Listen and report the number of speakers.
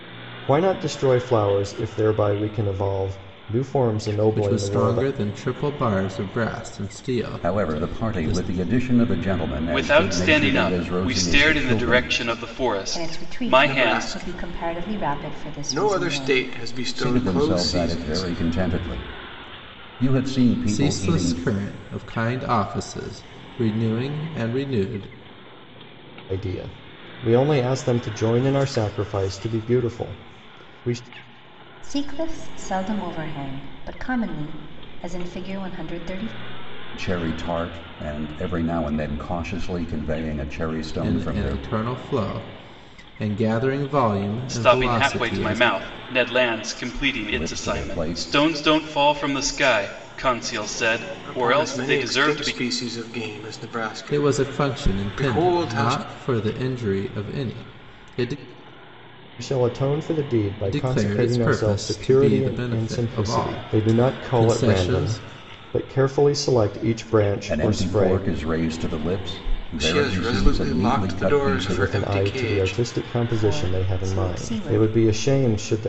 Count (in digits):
6